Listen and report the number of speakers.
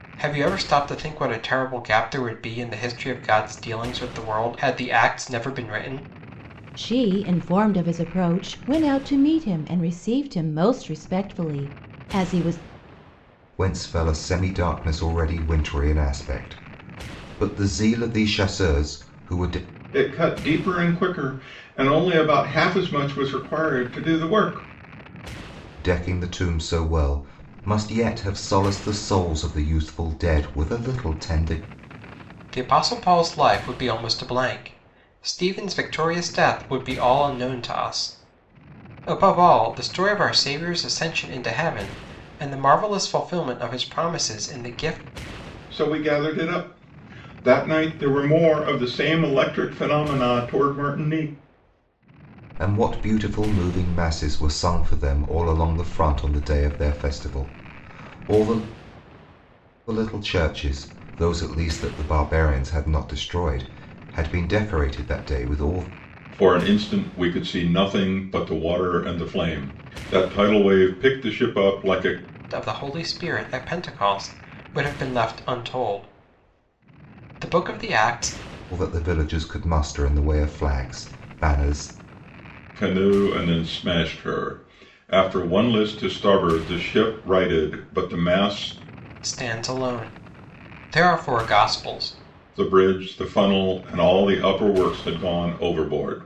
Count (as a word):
four